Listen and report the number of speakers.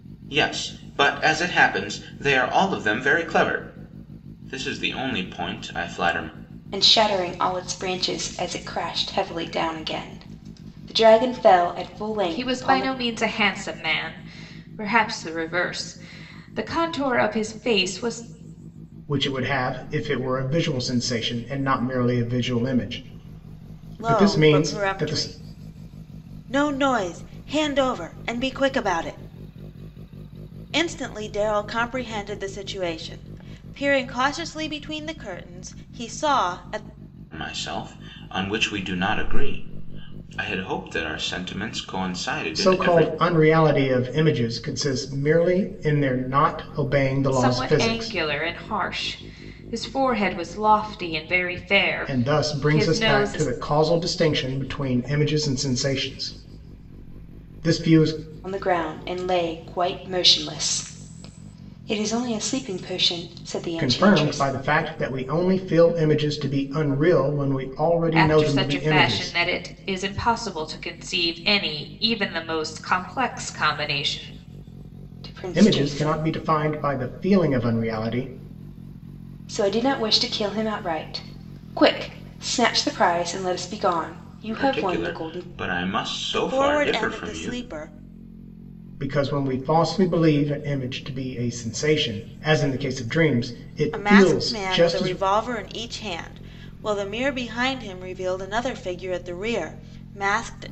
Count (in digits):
5